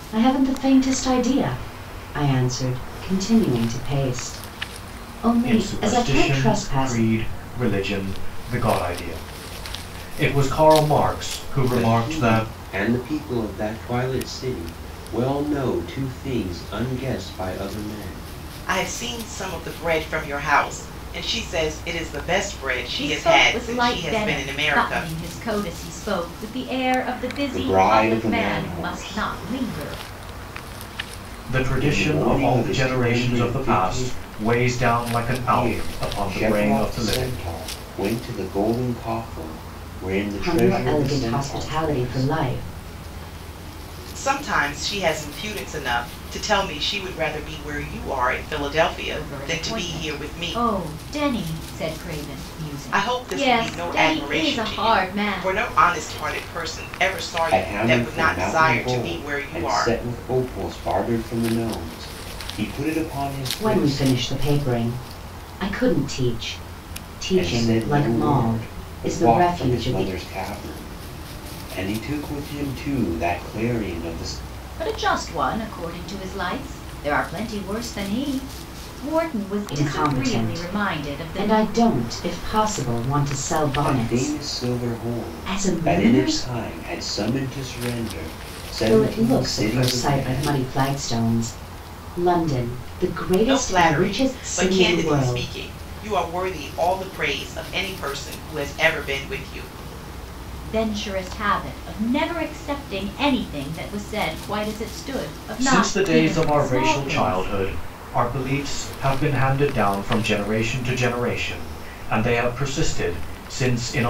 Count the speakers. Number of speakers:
5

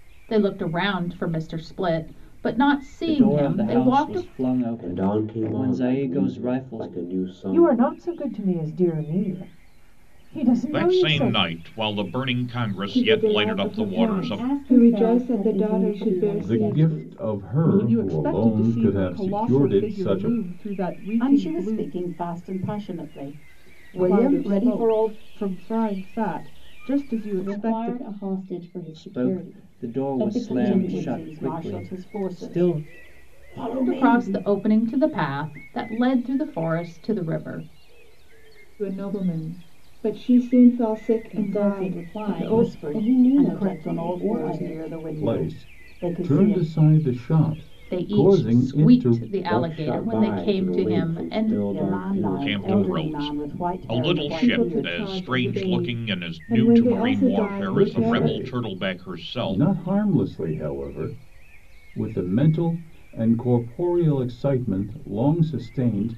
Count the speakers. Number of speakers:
10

